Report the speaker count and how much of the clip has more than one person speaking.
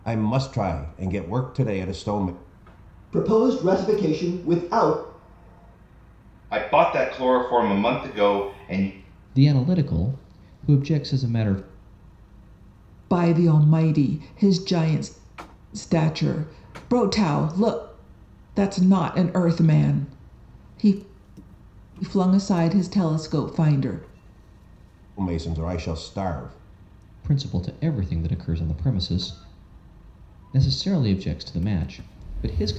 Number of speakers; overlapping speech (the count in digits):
5, no overlap